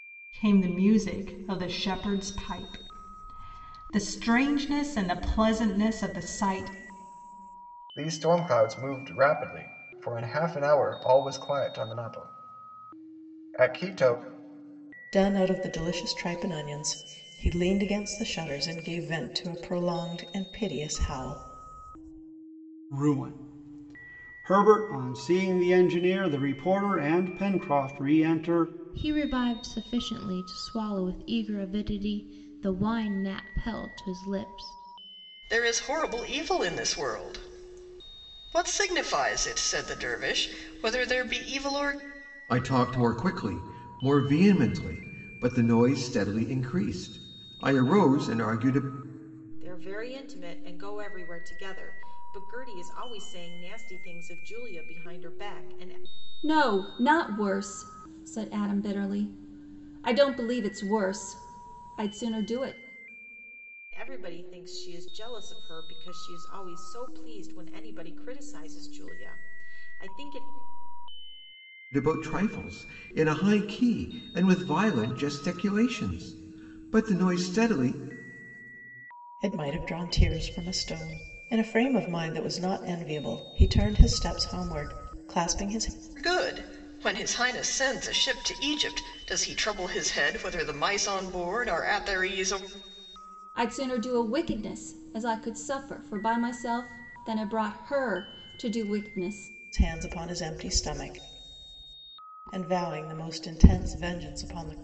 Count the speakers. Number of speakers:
nine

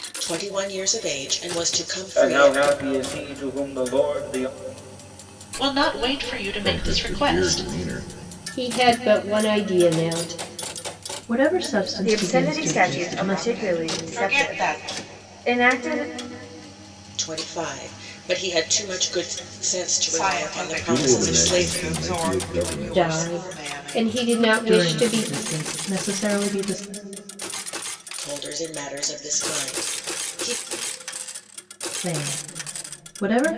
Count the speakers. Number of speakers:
eight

